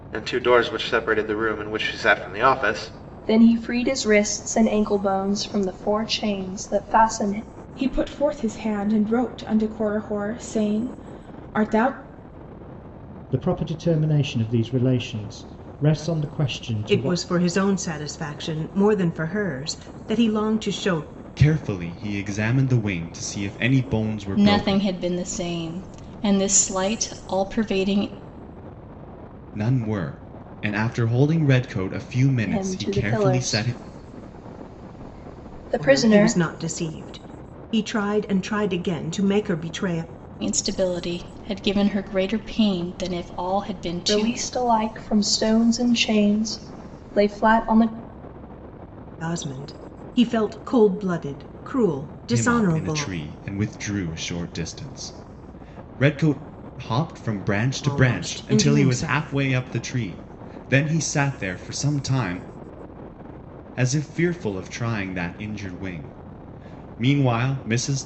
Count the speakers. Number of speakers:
7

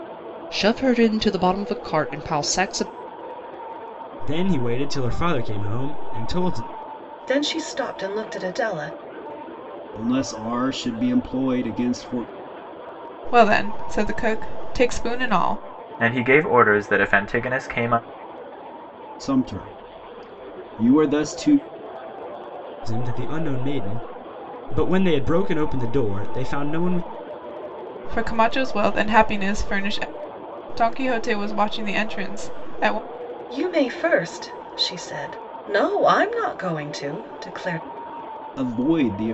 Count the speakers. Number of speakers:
6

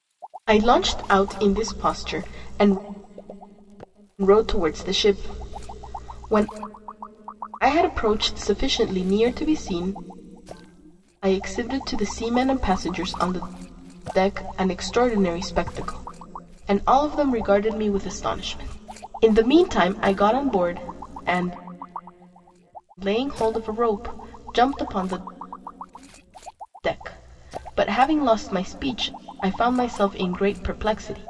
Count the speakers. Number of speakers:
1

